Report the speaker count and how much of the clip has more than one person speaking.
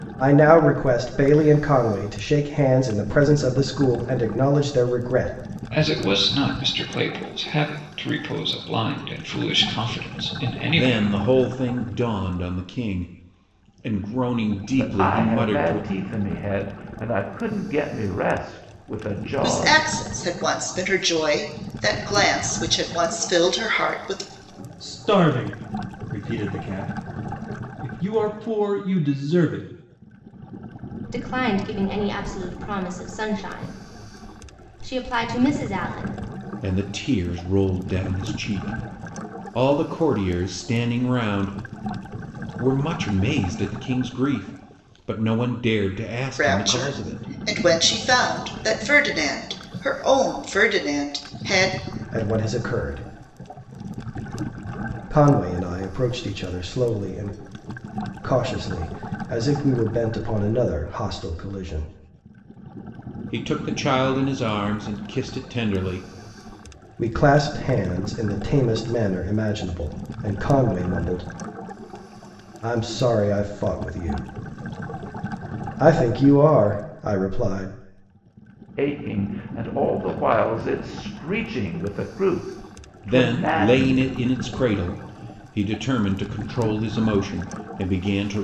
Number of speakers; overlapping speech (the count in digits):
7, about 5%